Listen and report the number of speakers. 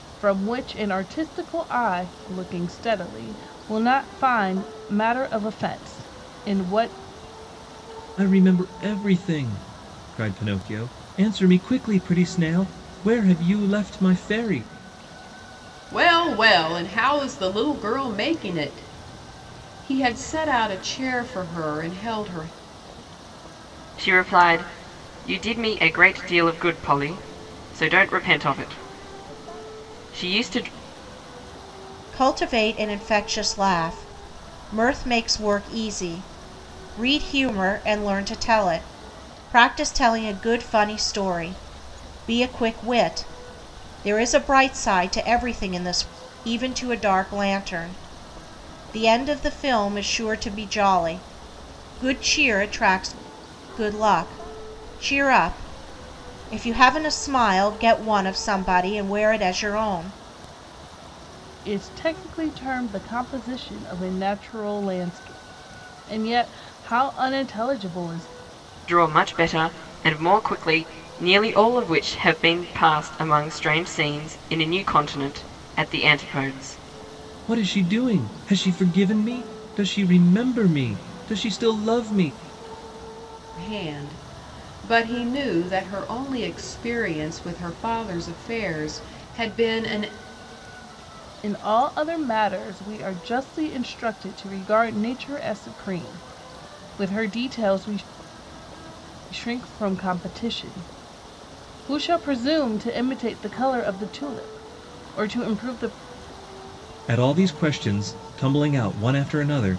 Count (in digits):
5